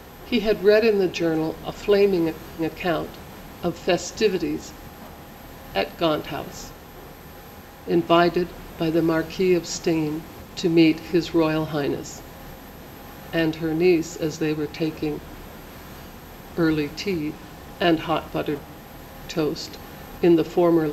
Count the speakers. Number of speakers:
1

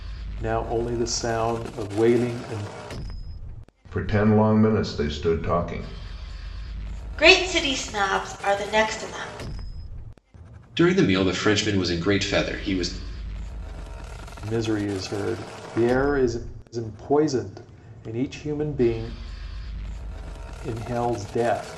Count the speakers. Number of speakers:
4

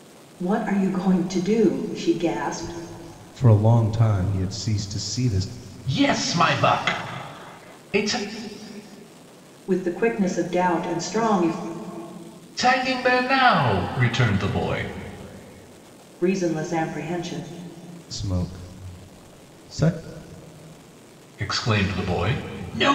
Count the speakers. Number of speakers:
3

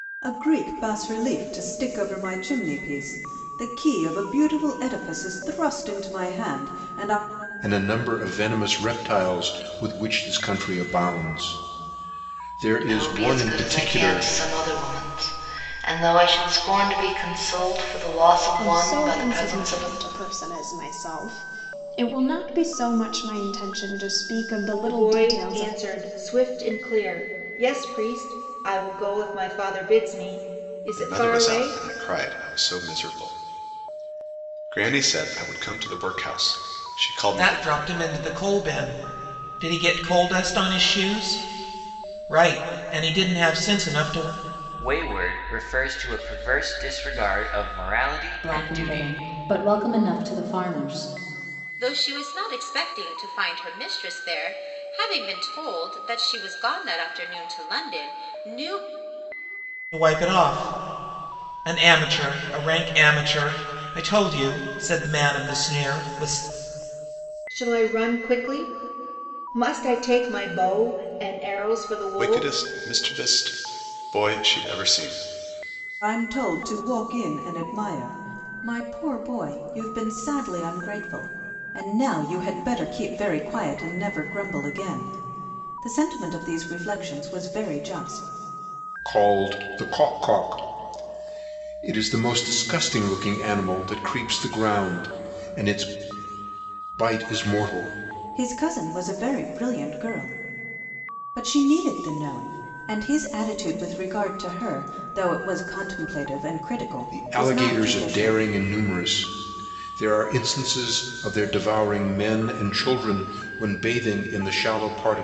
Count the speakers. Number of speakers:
10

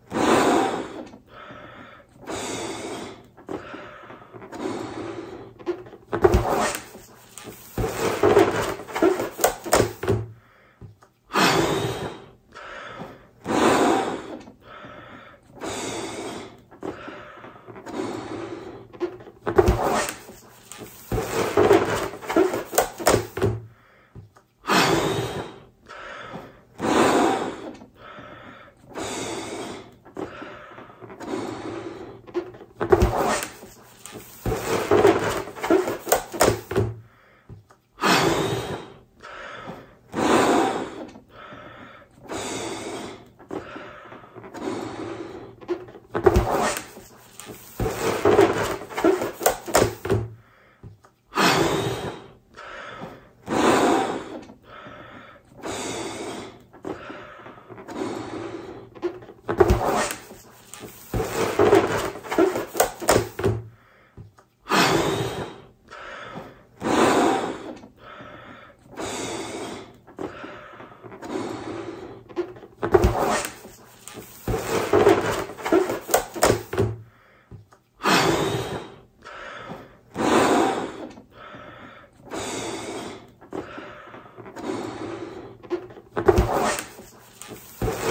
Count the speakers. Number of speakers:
0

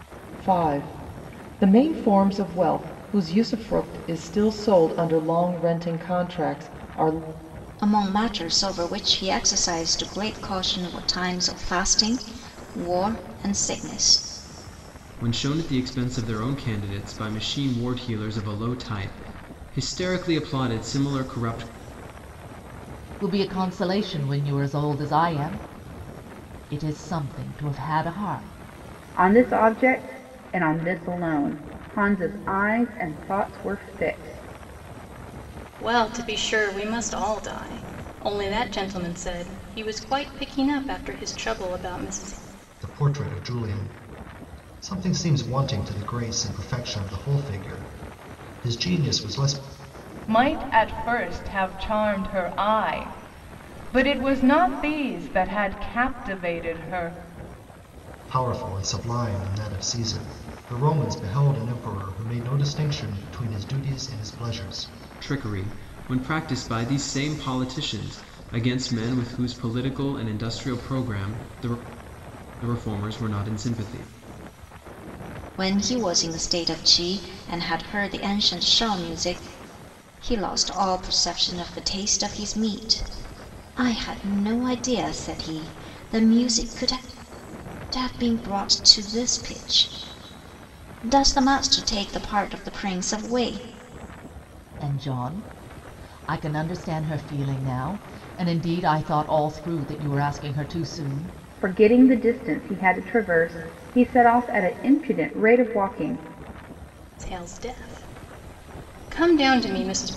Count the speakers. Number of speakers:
8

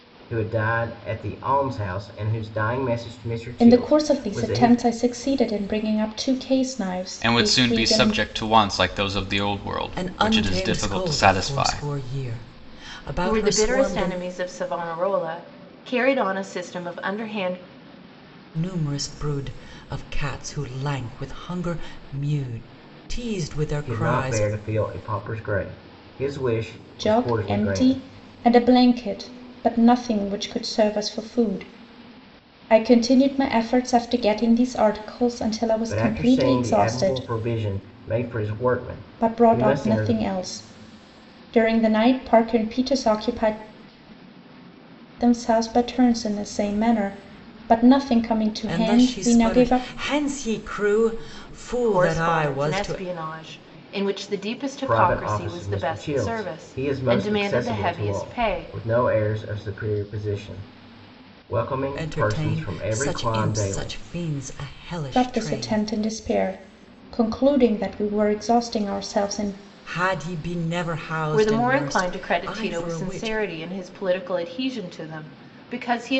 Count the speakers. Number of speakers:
5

